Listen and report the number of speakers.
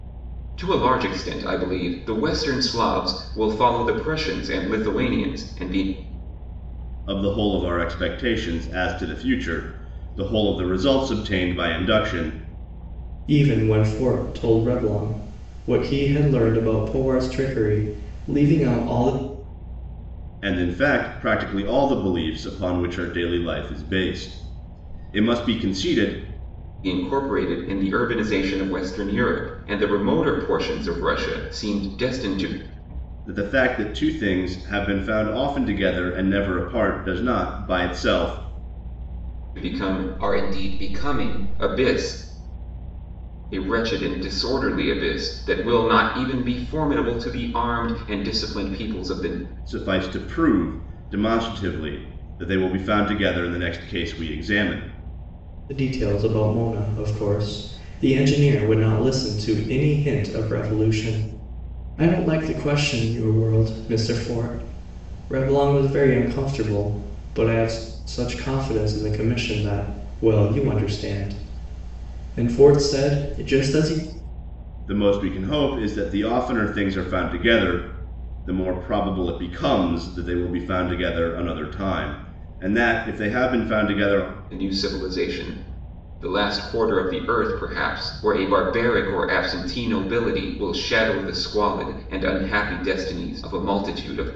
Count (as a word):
three